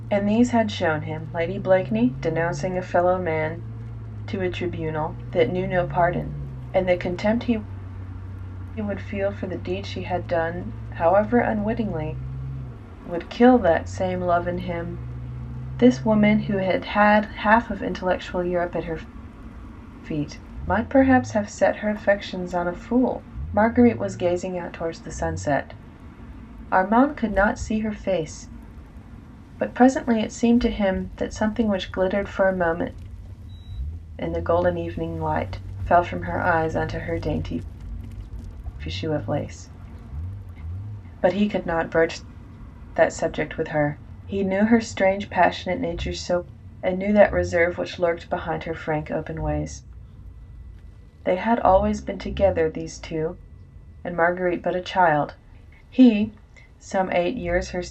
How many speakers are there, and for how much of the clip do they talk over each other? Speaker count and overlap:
1, no overlap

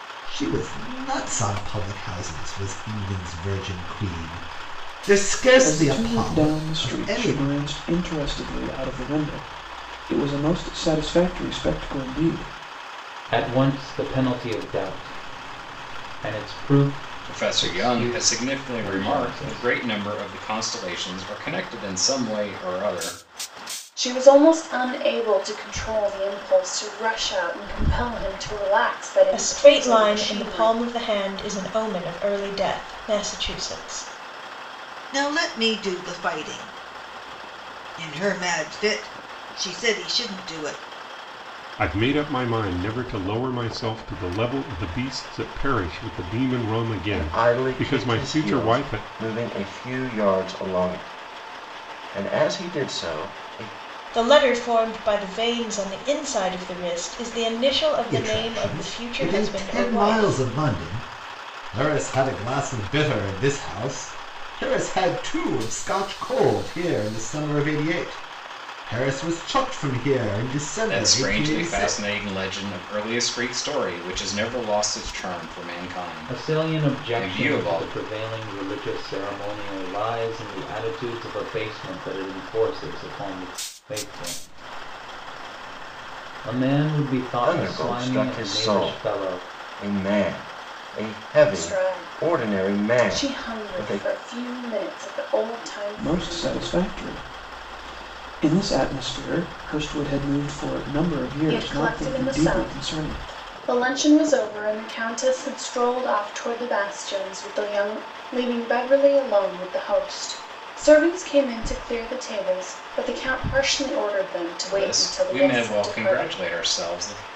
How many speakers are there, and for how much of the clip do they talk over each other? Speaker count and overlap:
9, about 19%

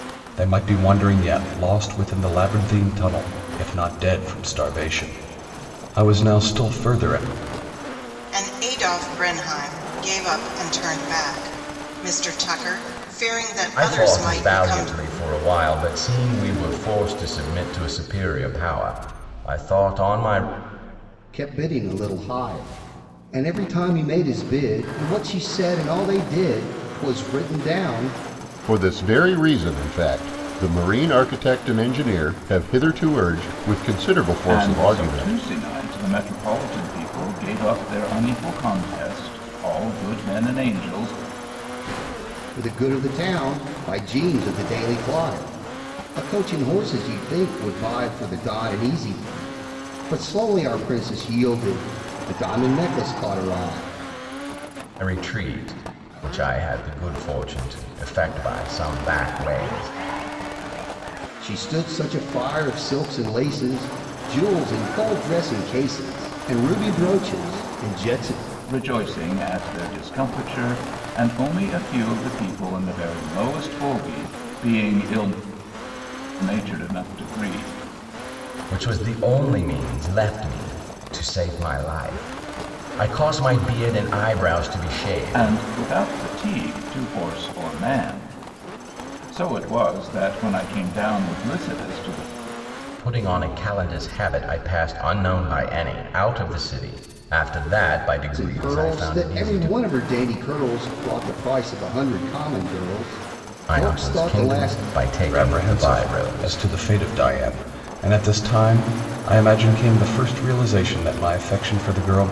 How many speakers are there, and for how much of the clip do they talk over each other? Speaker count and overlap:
6, about 6%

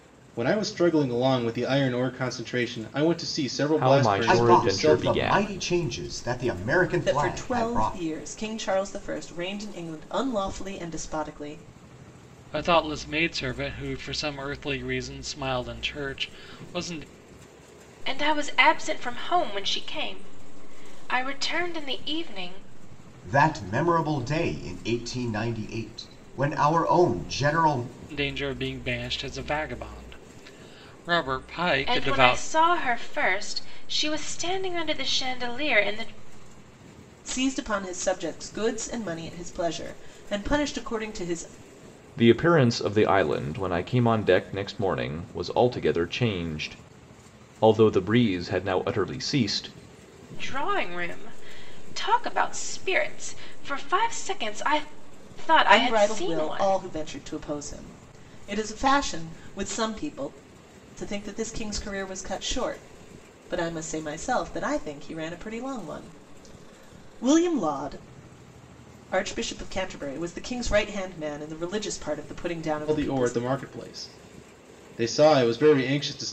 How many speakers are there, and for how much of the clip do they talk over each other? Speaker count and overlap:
6, about 7%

